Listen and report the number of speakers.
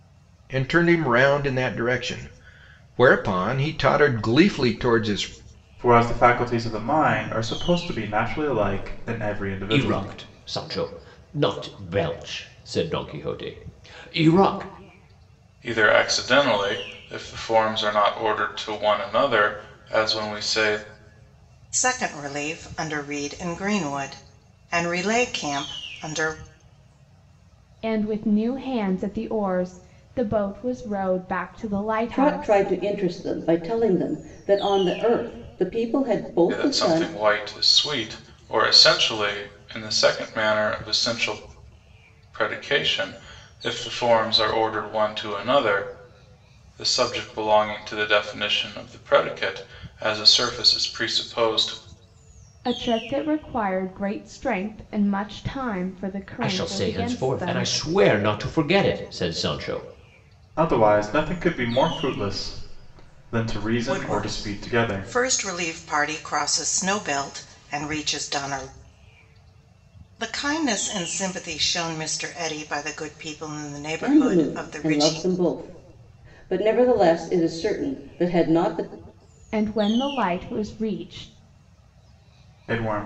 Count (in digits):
7